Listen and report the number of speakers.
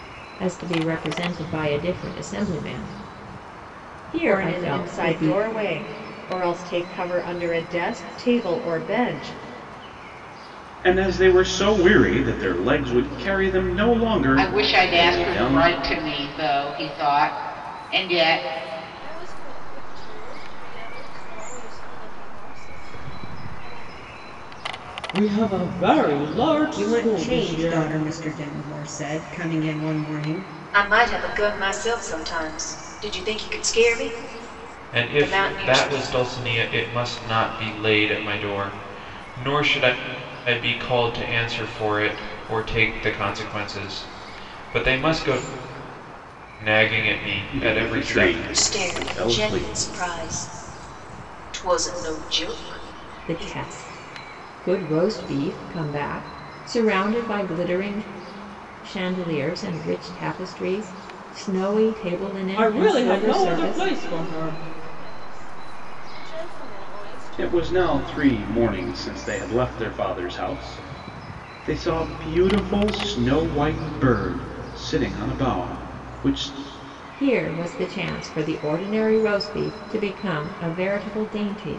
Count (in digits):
9